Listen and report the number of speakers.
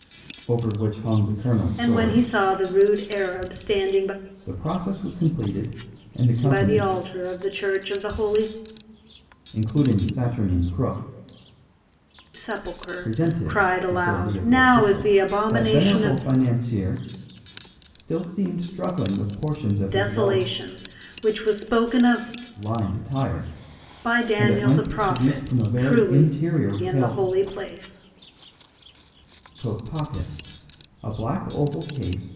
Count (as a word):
two